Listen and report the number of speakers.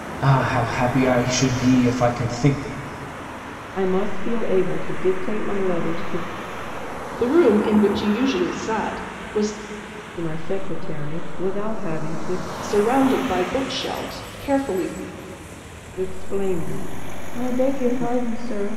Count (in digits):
3